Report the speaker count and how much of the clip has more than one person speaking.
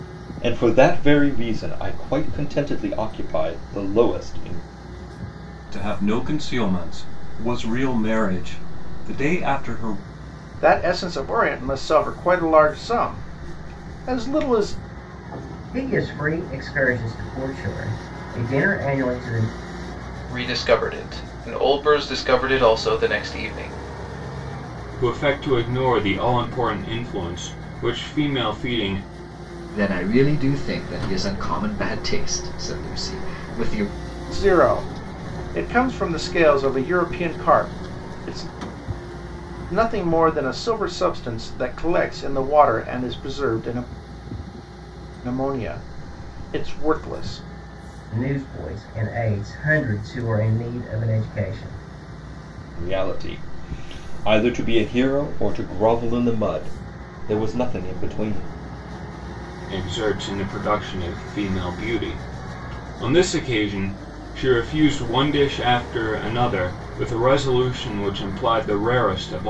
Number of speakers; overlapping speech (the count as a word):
seven, no overlap